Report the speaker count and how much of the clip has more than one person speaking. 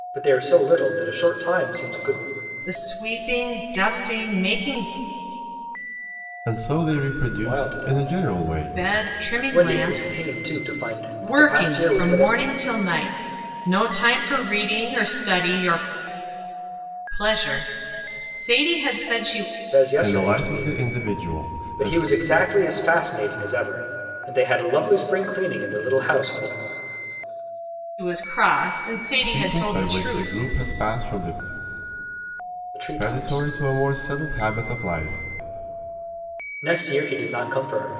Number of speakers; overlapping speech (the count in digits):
3, about 18%